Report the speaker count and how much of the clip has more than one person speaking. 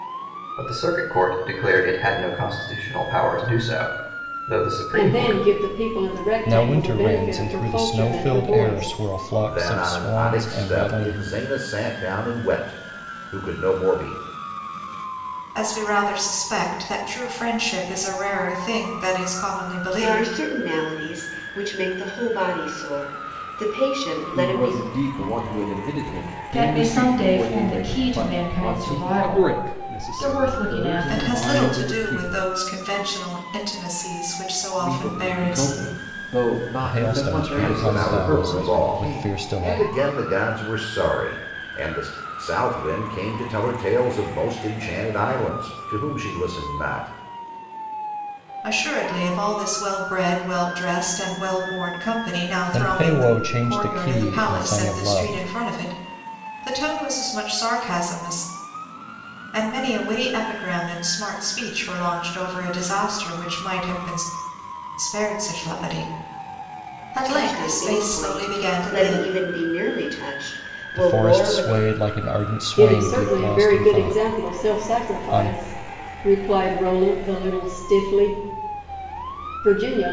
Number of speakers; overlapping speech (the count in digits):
9, about 31%